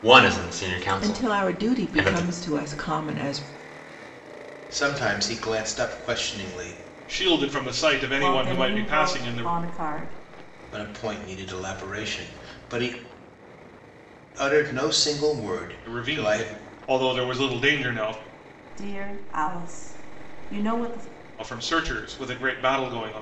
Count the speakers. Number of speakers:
five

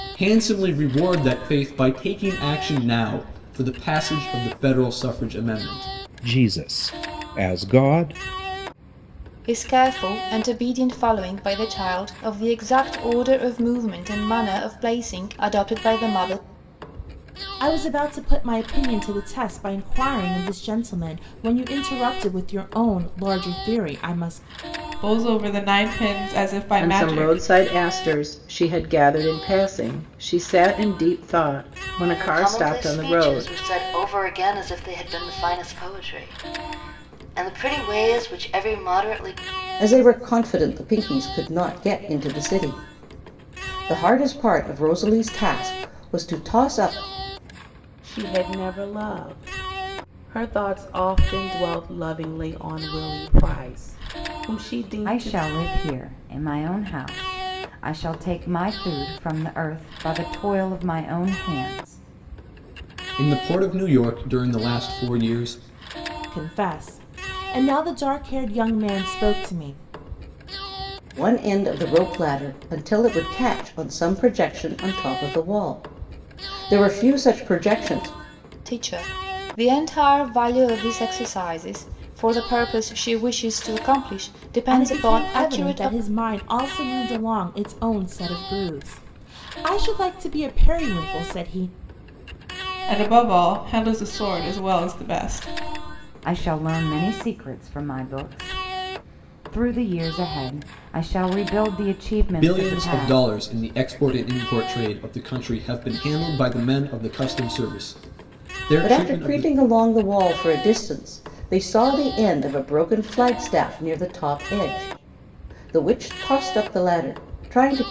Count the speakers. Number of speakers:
ten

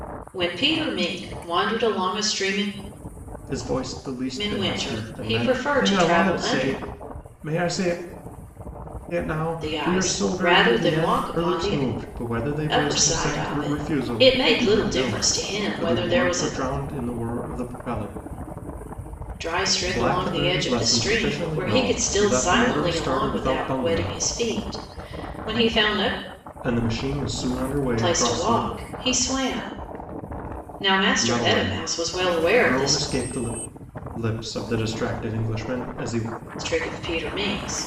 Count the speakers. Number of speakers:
two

